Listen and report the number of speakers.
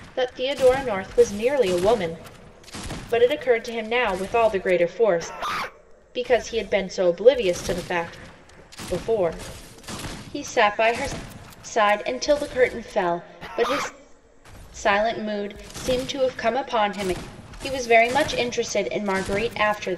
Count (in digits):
1